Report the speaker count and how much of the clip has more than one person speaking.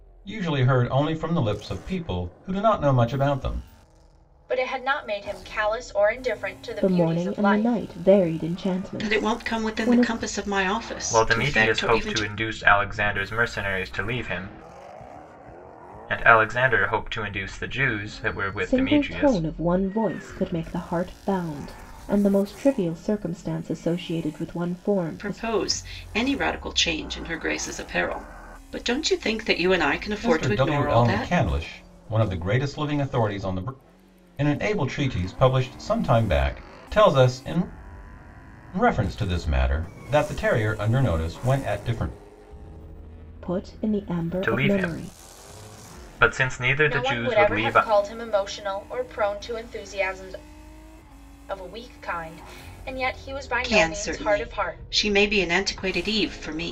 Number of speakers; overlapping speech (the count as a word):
five, about 16%